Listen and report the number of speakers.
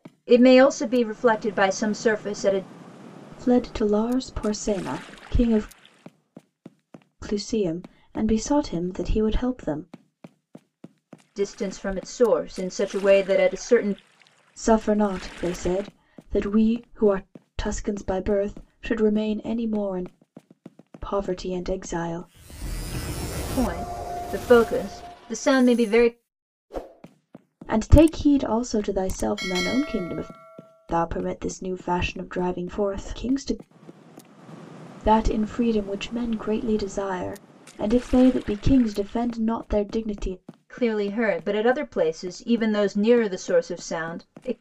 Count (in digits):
2